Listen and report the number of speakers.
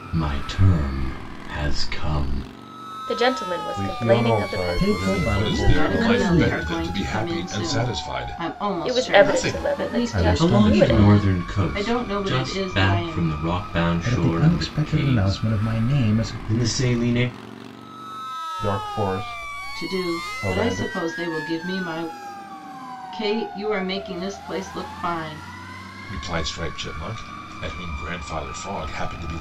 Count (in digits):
6